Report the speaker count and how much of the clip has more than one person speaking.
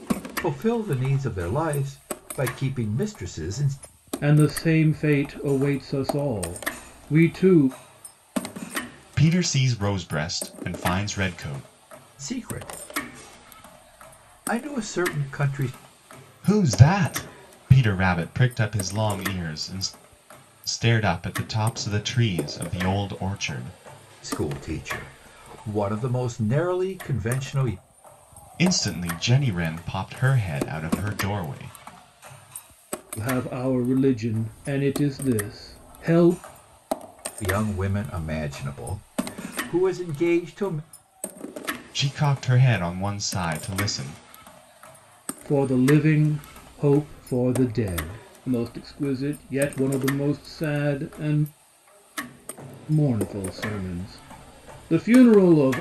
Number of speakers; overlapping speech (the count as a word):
three, no overlap